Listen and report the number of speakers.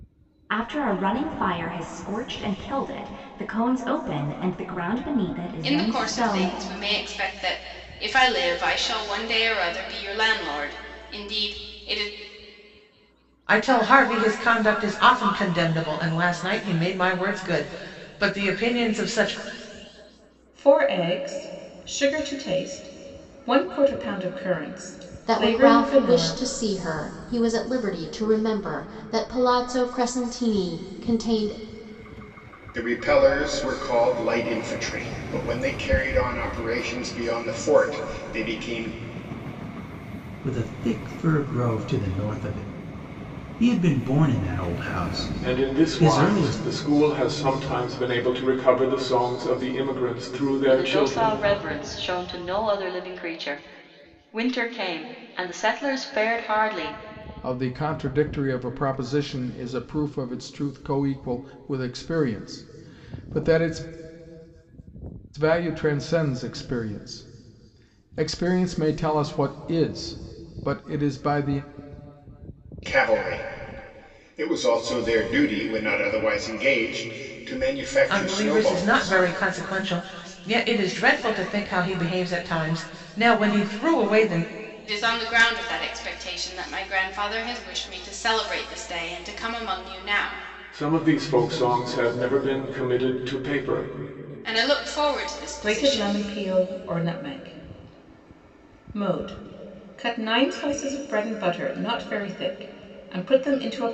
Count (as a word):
ten